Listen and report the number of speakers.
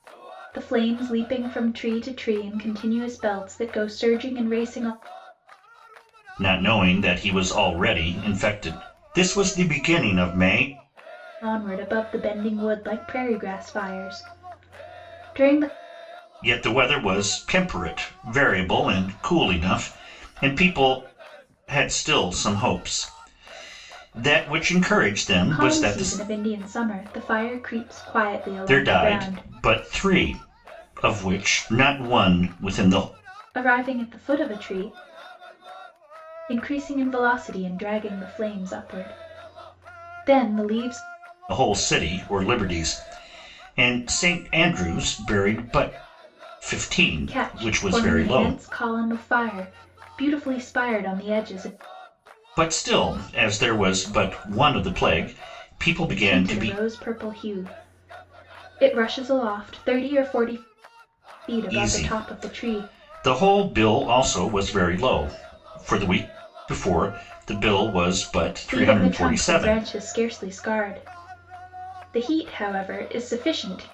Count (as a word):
two